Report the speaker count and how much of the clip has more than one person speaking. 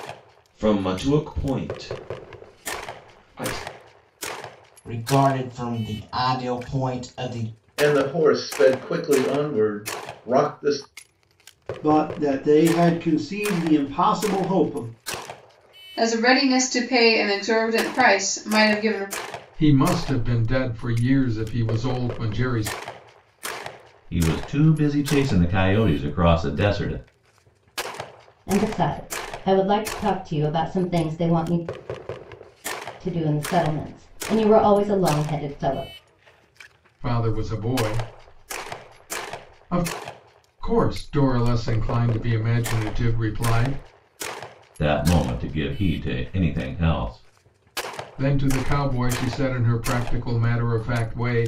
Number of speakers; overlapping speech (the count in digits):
8, no overlap